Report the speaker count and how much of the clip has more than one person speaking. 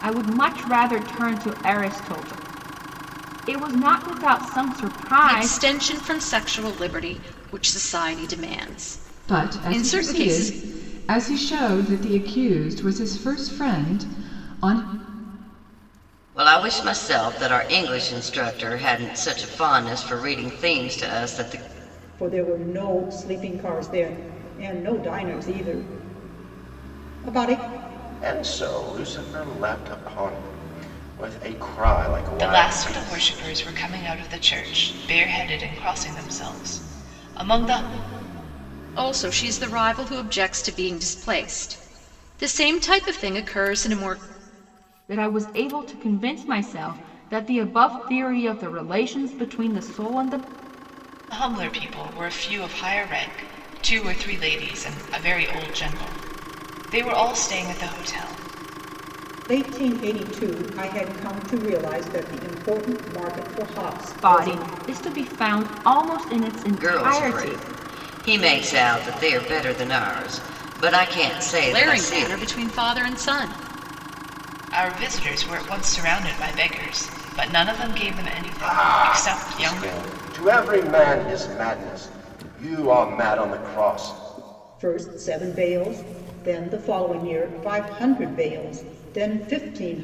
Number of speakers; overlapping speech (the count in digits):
7, about 7%